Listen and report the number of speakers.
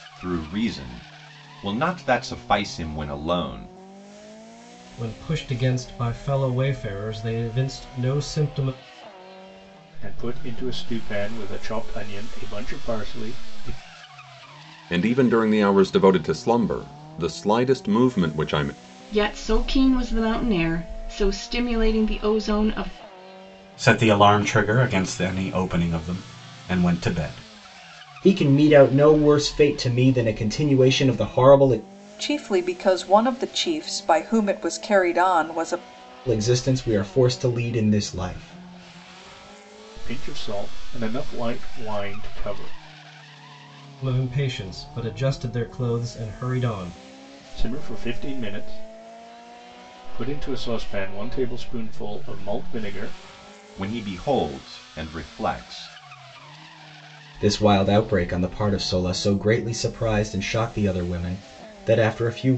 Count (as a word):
eight